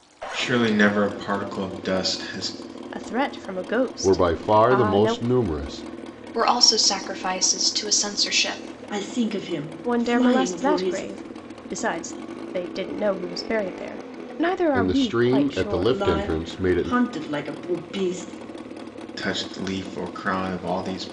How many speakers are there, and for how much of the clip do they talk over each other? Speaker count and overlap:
5, about 22%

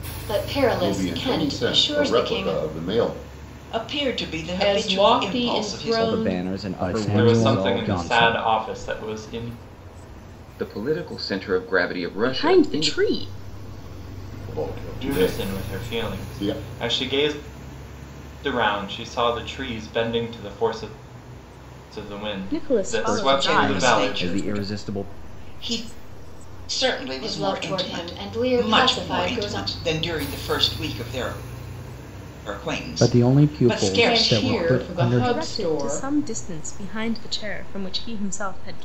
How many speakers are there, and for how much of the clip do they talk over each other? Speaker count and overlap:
9, about 41%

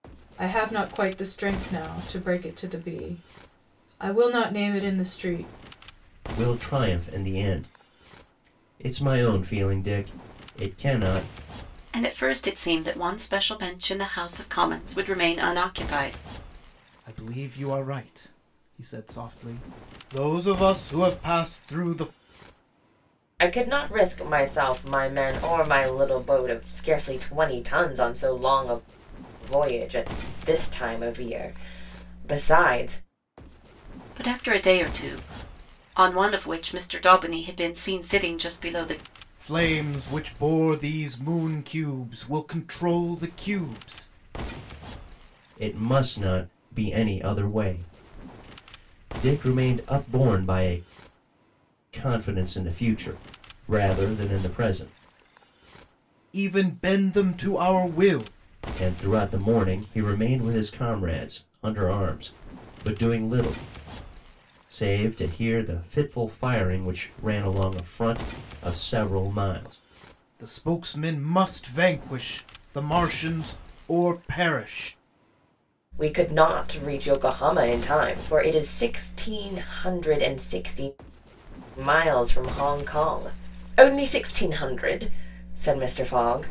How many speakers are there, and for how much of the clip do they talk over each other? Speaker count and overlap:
5, no overlap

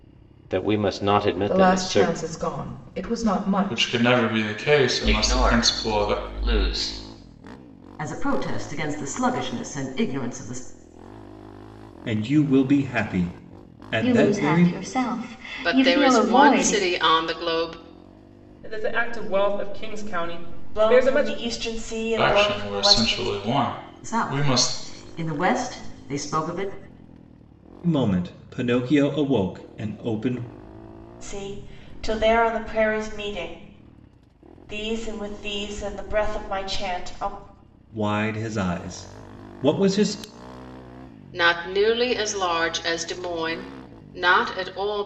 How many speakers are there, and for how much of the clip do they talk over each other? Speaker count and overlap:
10, about 15%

